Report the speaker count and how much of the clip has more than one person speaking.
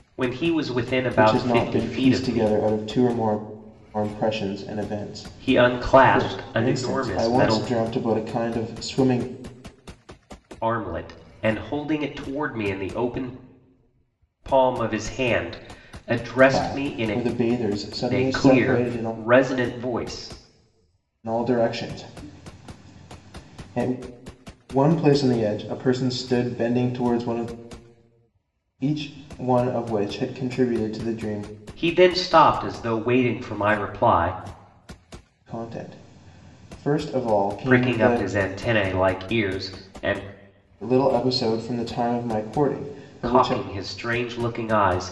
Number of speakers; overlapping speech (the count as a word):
two, about 14%